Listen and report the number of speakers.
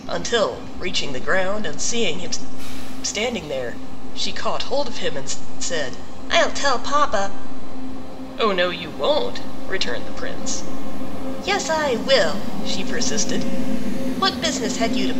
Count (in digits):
1